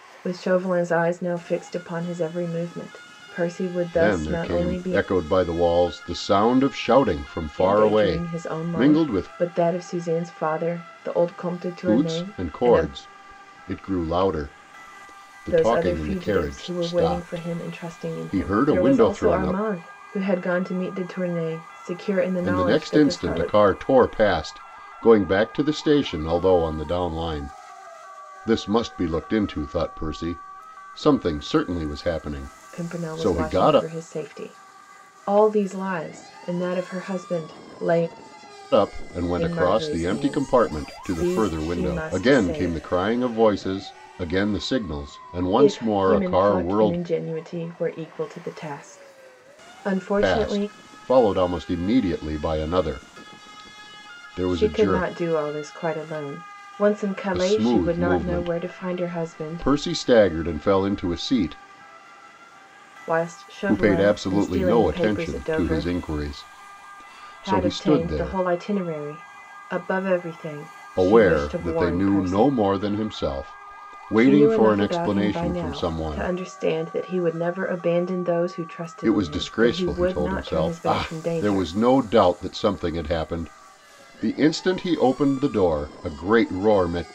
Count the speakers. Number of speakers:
2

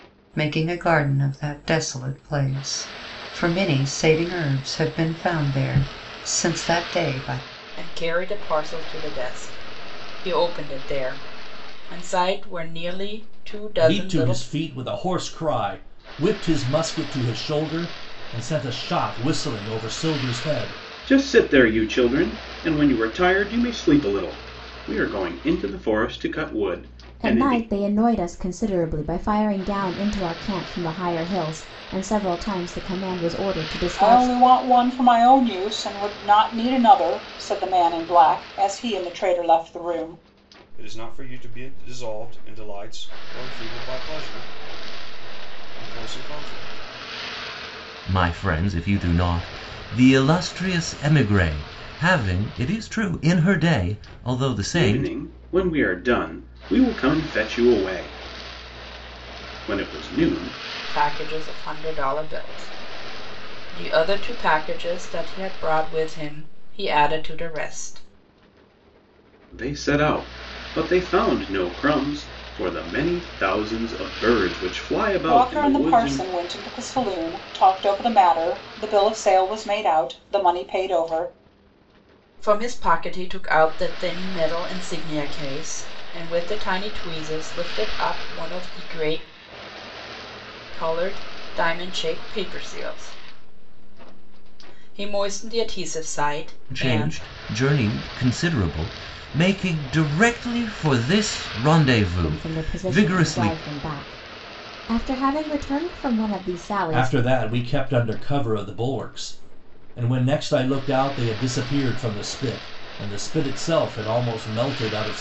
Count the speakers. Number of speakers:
8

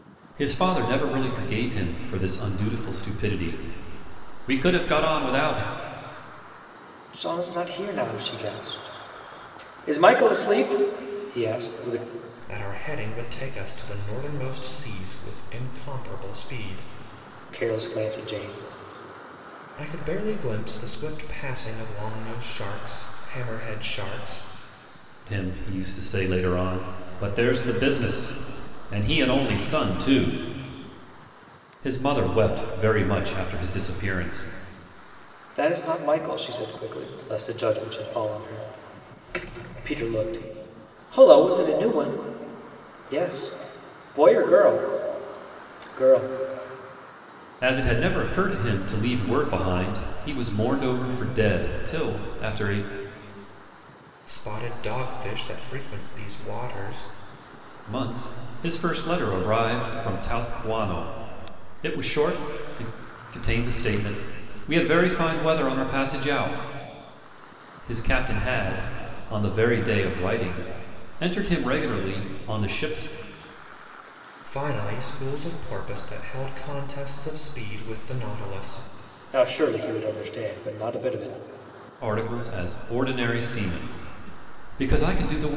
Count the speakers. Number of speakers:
3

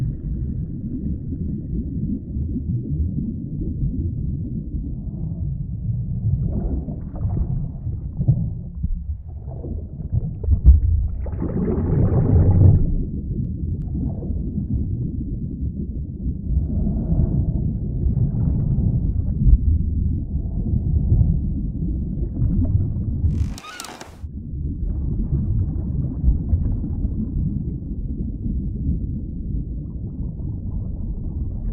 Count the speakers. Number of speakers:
0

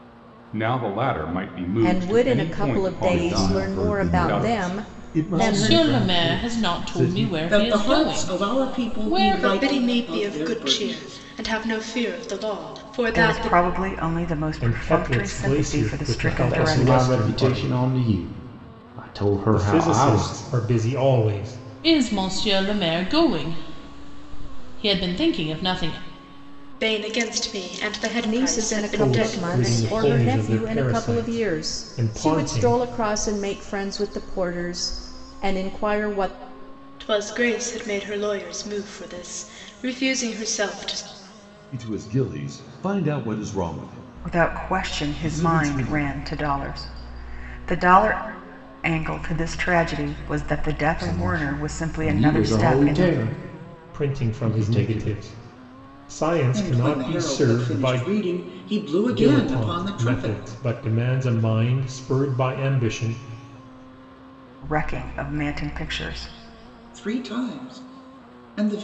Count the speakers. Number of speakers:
9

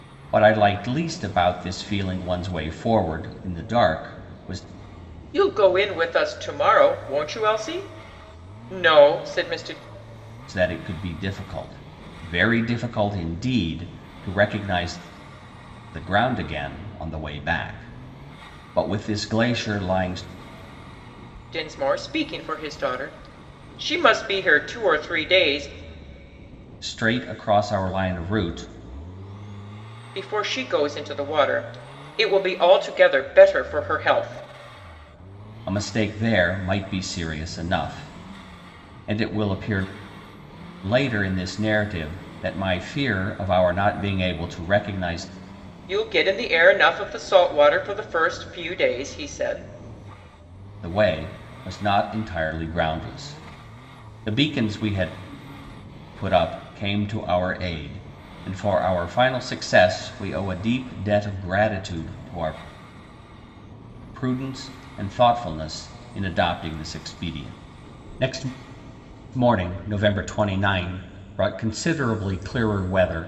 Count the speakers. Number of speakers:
2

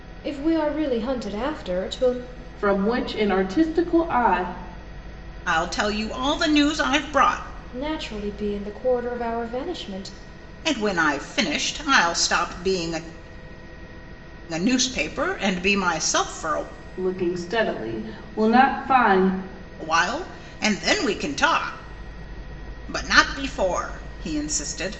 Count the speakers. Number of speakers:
3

